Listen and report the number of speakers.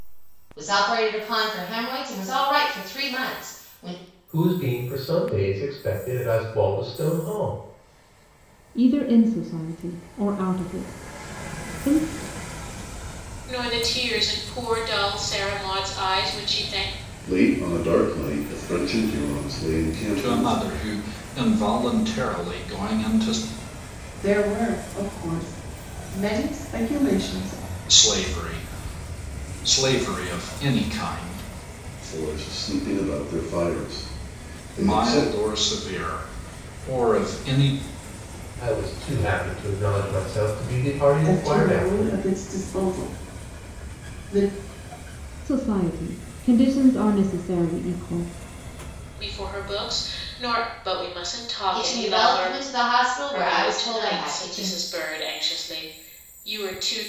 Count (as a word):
seven